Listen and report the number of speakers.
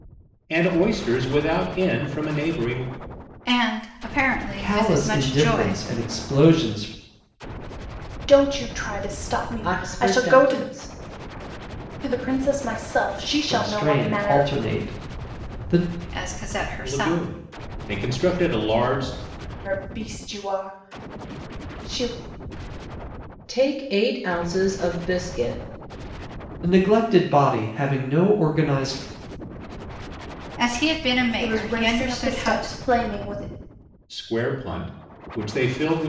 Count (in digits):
5